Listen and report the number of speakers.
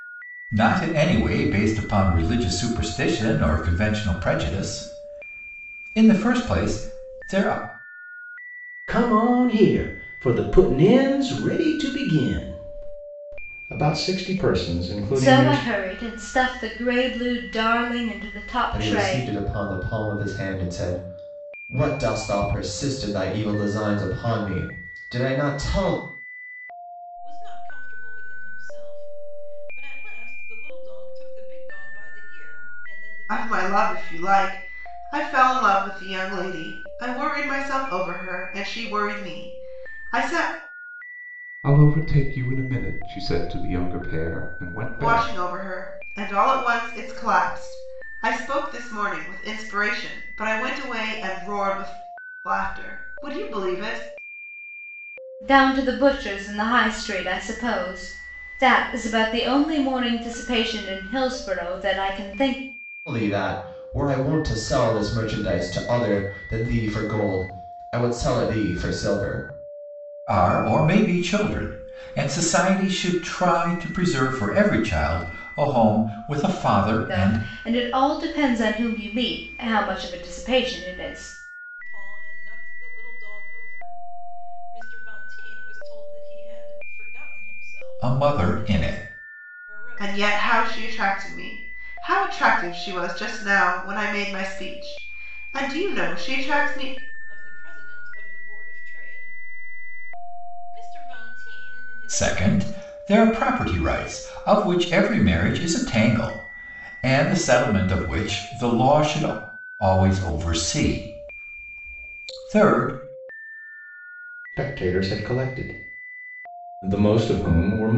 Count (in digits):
7